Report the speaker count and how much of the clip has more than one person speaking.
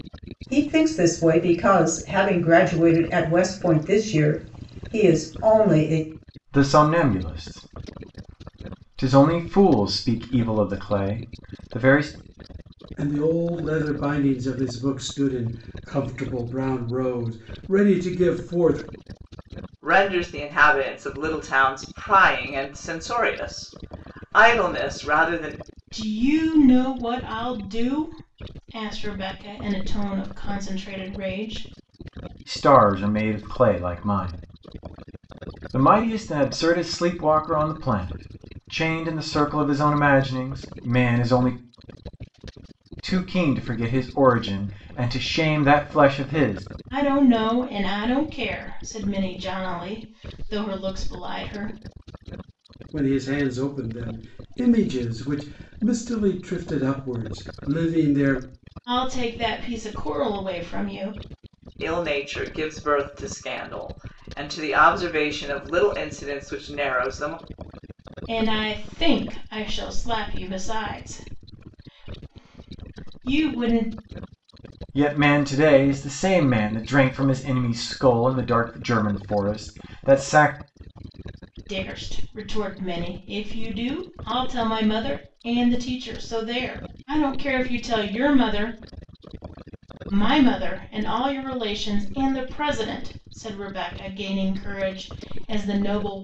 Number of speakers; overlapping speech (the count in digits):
5, no overlap